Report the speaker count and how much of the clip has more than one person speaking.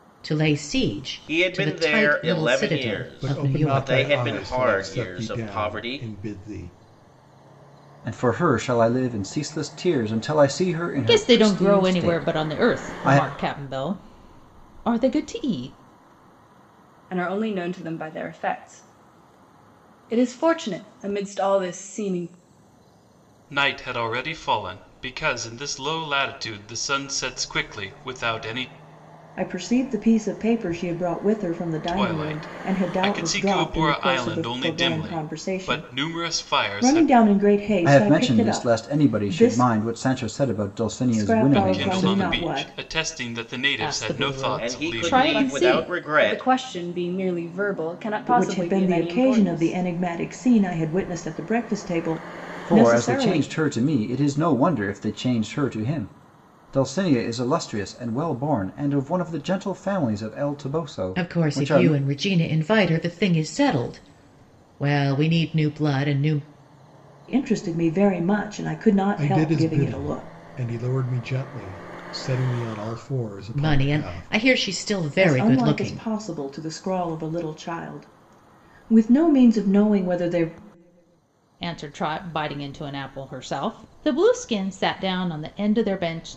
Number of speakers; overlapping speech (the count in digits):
8, about 29%